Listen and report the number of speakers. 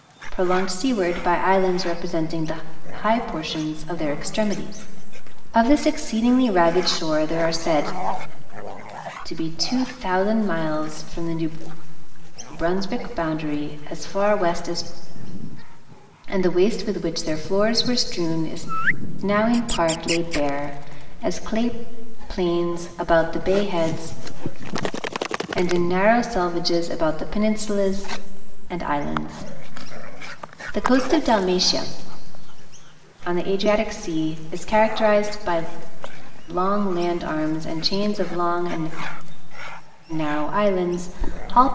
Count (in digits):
1